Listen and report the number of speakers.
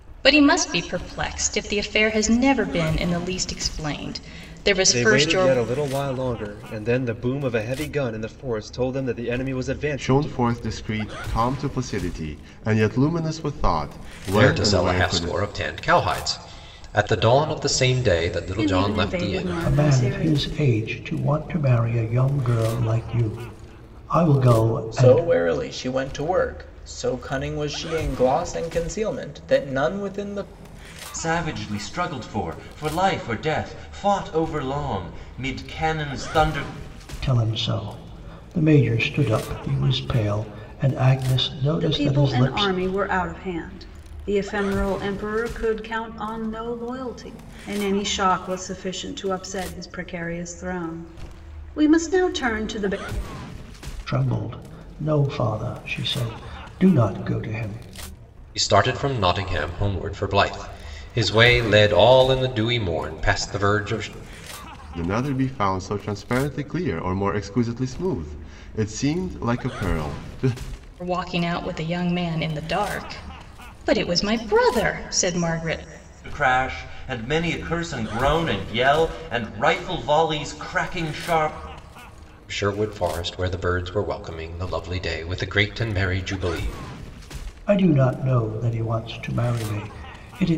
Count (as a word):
eight